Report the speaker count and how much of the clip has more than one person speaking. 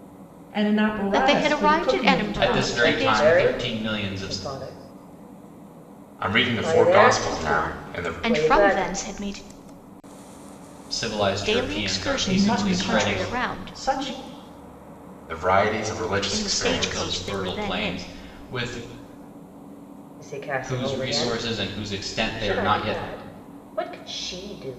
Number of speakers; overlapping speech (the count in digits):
5, about 46%